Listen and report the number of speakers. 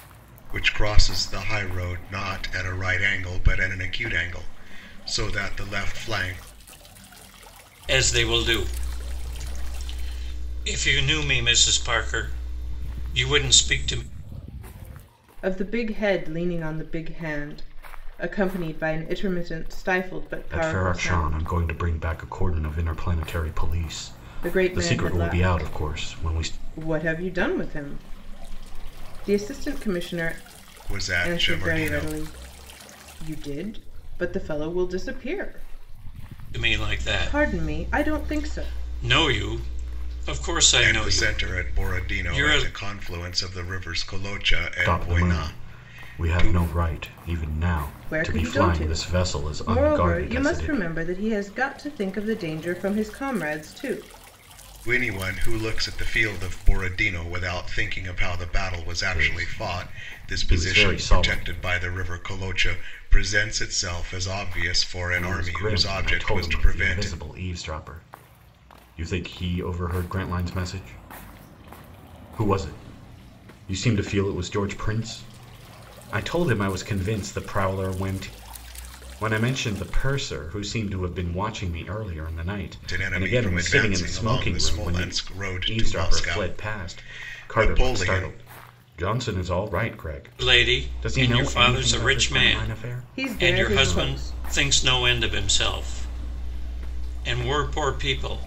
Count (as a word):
four